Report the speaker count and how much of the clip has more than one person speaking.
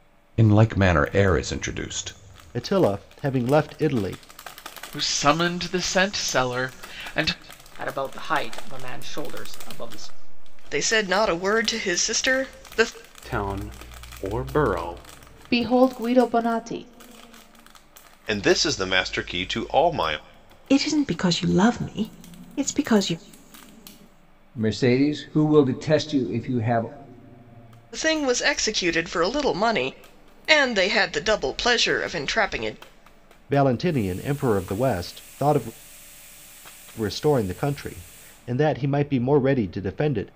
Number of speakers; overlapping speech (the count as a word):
ten, no overlap